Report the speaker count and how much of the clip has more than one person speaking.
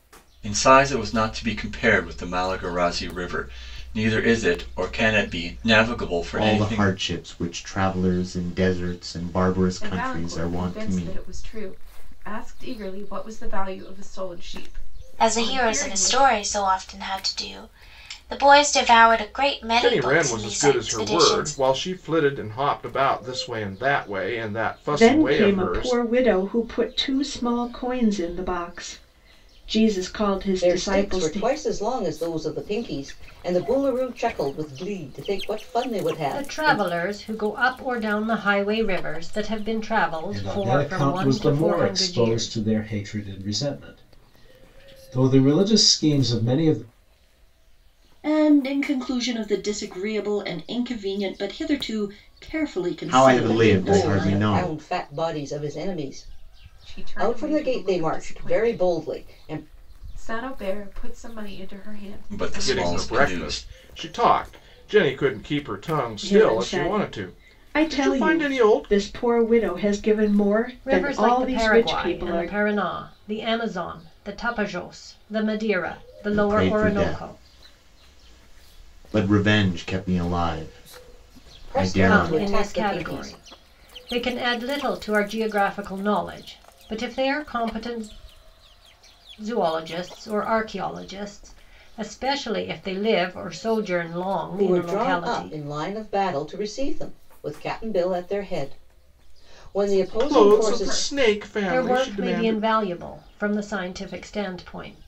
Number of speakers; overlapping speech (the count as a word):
ten, about 25%